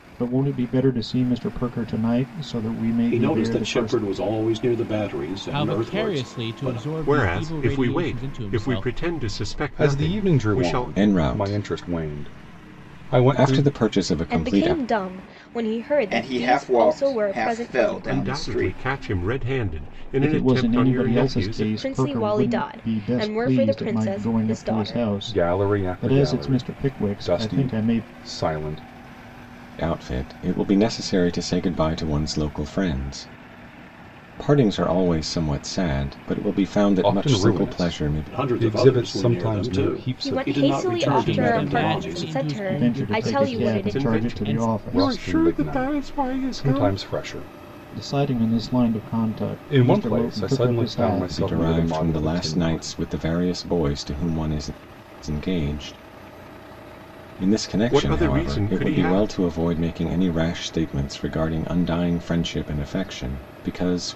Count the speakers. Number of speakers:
8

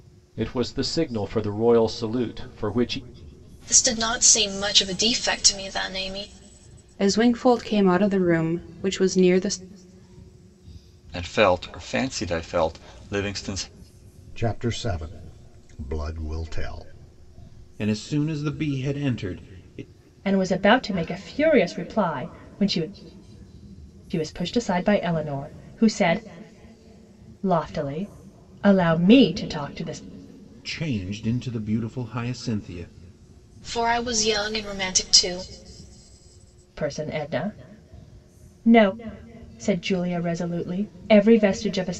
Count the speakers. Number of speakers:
7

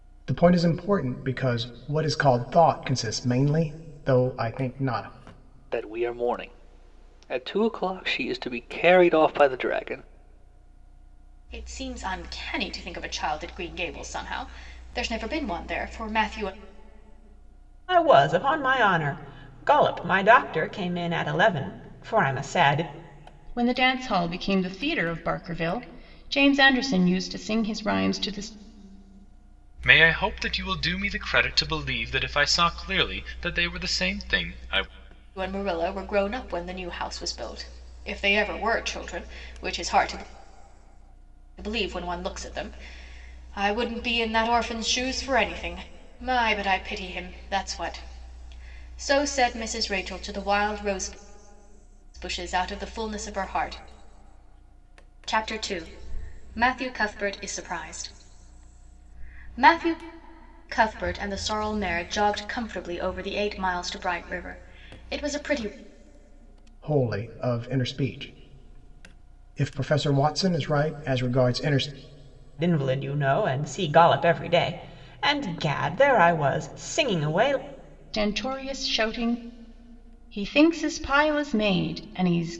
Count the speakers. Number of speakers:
6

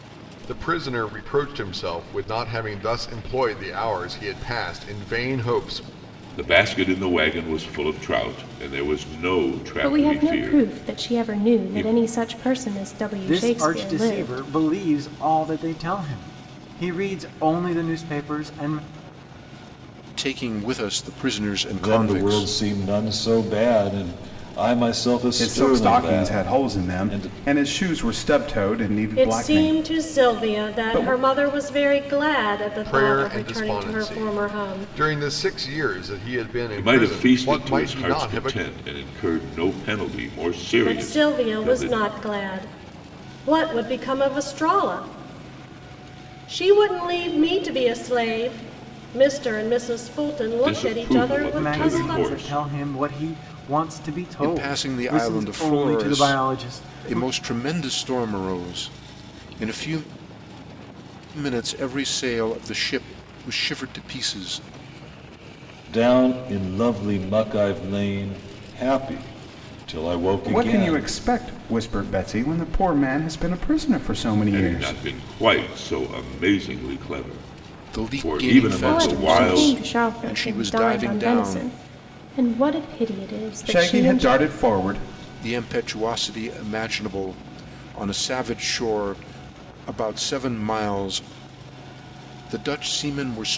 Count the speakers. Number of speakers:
8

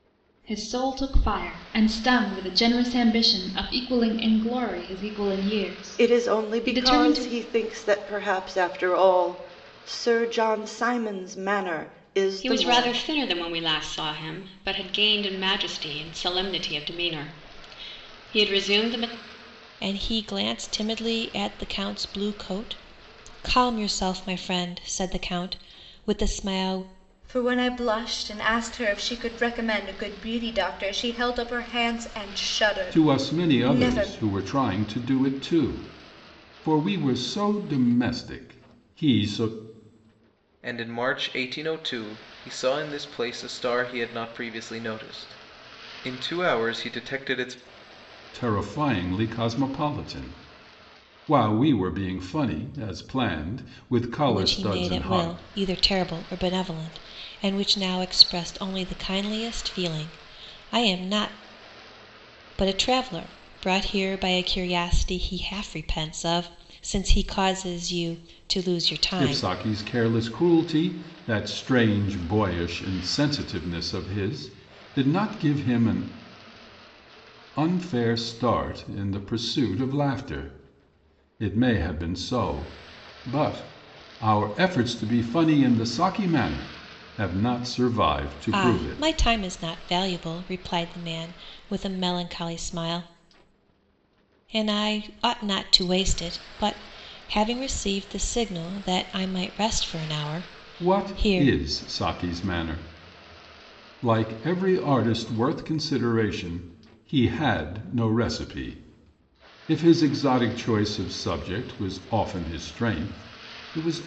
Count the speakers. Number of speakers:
7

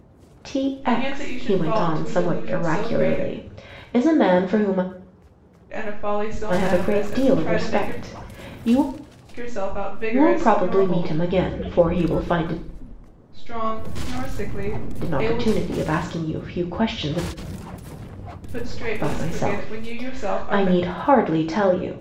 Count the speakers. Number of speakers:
2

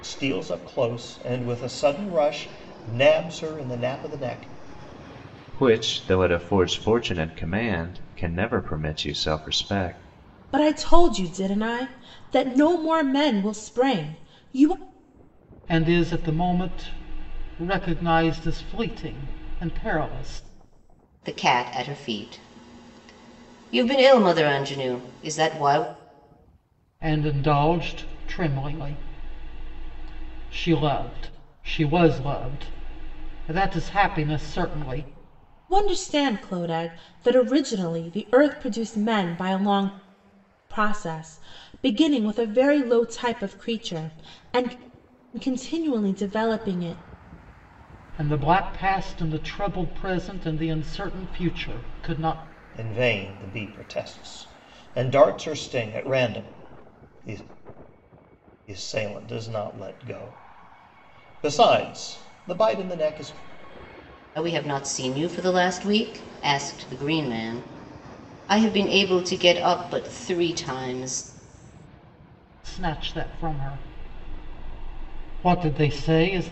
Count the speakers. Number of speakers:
5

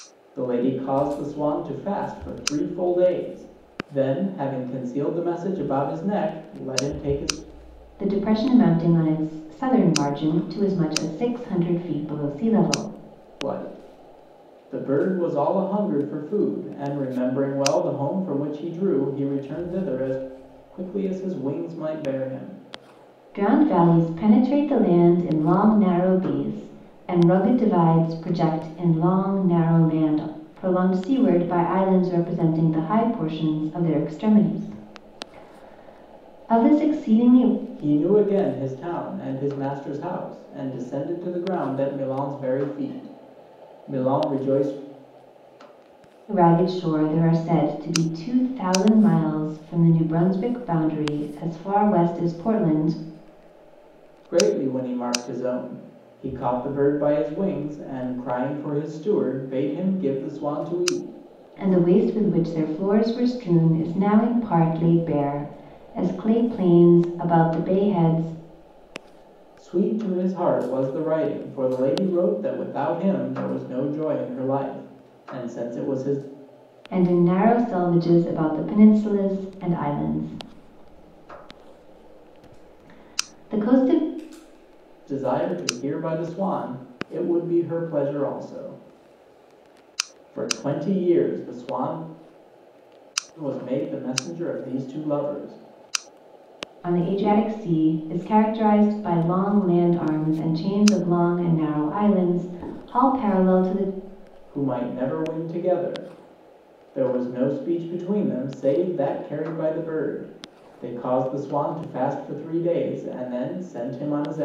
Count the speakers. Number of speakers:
2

